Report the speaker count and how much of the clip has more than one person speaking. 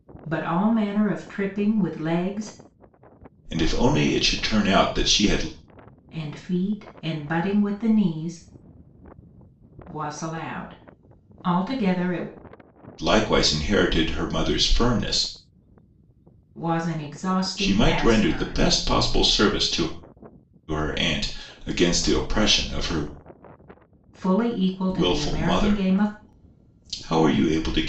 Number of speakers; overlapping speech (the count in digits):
2, about 9%